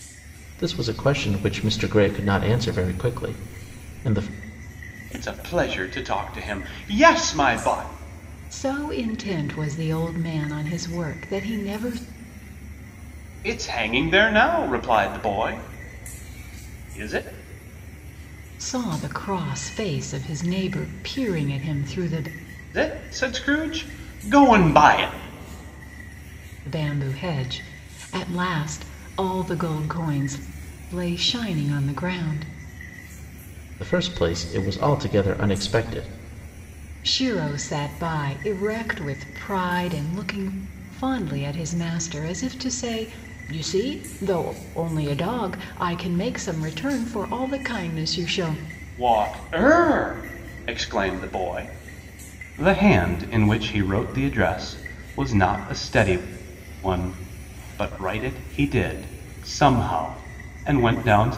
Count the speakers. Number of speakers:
three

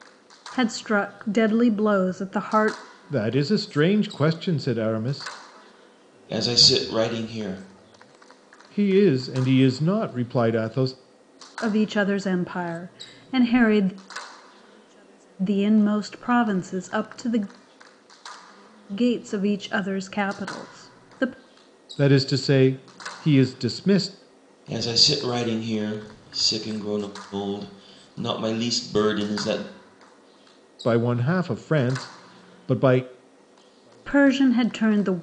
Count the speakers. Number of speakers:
three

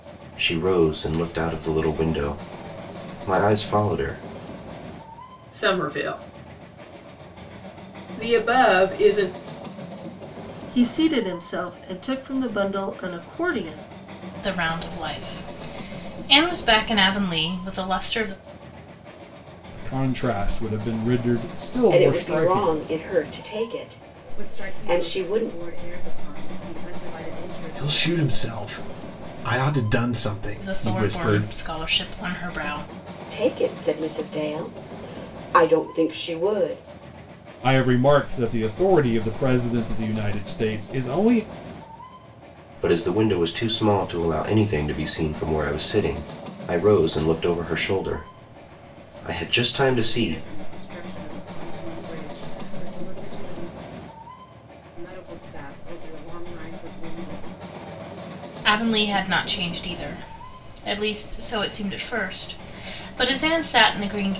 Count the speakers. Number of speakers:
eight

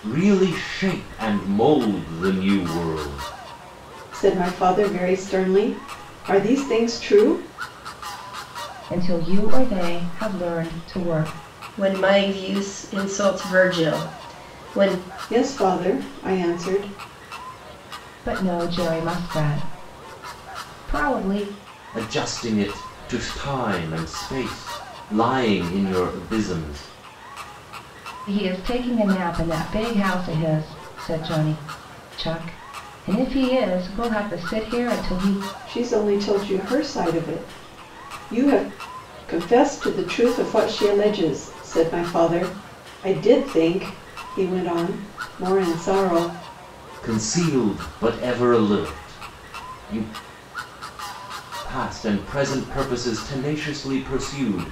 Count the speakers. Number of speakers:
four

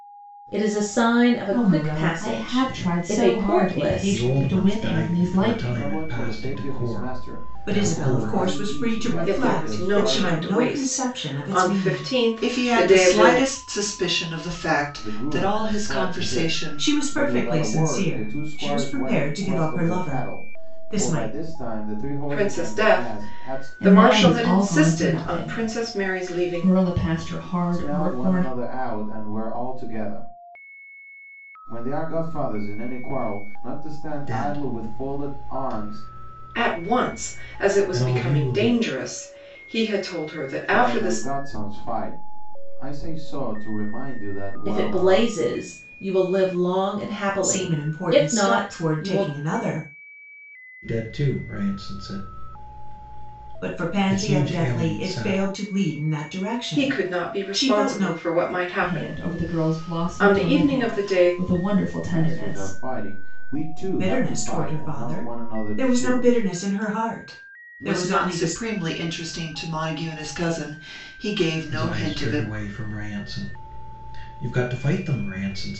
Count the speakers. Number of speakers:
seven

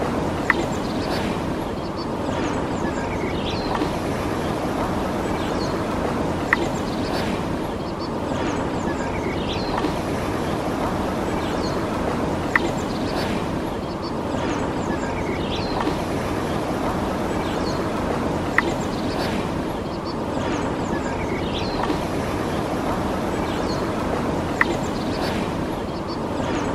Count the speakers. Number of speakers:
zero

